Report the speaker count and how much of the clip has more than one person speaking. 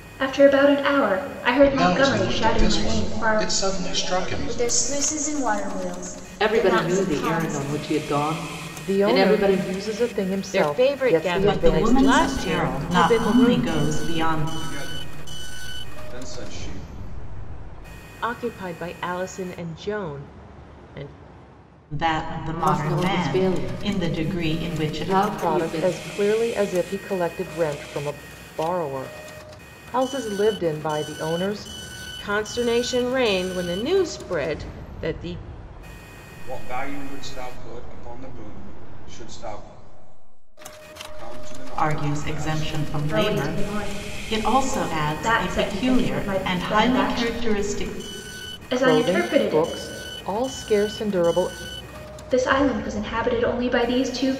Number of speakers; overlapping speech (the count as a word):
eight, about 38%